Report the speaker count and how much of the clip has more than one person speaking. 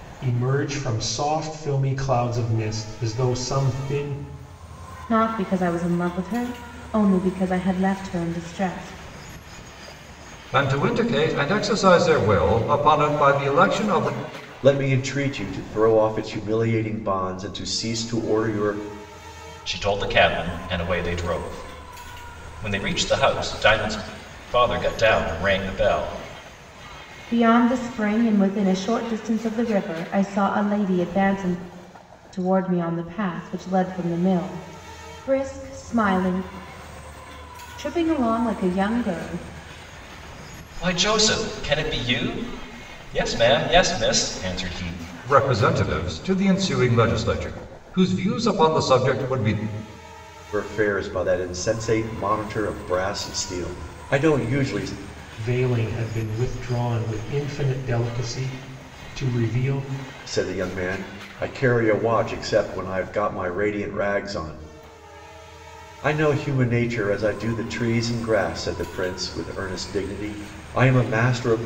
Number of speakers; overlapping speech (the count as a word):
five, no overlap